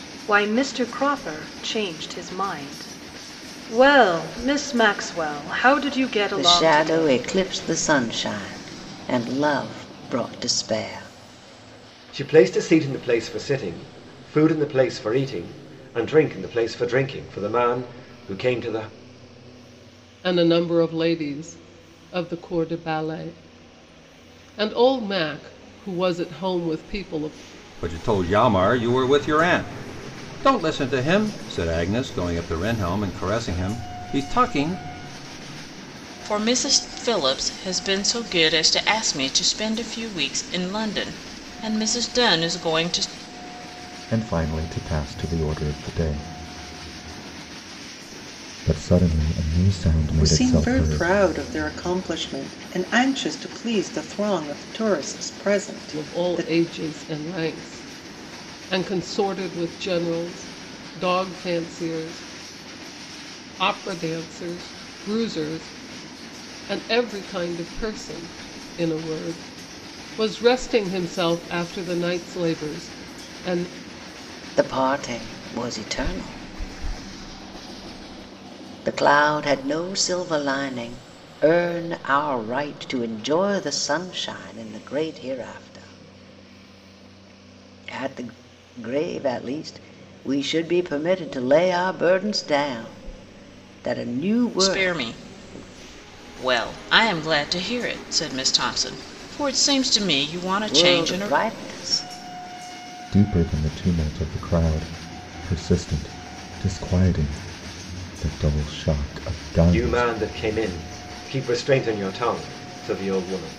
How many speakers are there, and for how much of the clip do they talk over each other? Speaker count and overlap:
8, about 4%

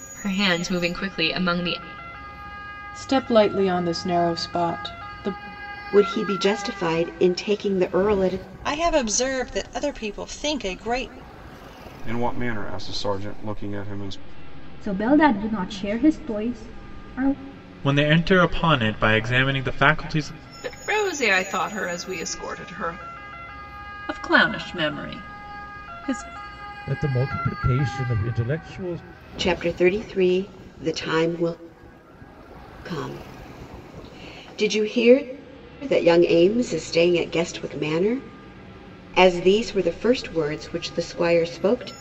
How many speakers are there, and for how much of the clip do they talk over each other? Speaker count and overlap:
10, no overlap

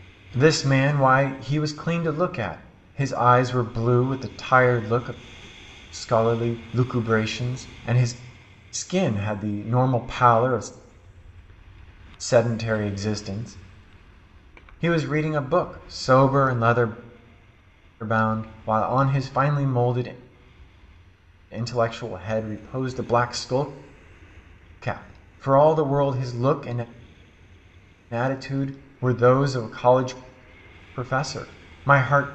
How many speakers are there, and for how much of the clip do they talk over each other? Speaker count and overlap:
1, no overlap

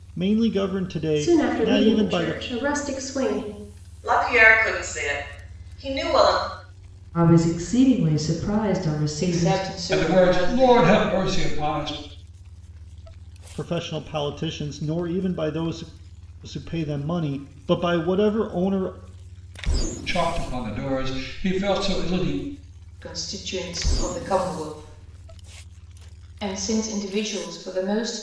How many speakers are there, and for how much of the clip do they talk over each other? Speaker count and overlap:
6, about 10%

